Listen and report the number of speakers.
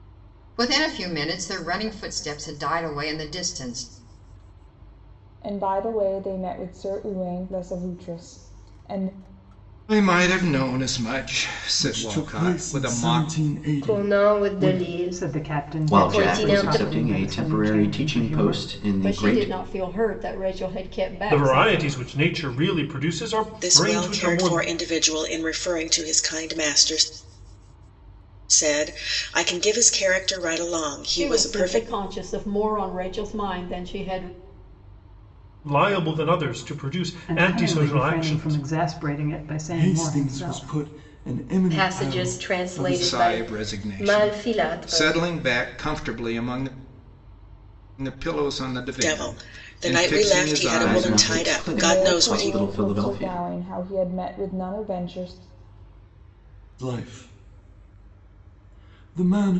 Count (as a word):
ten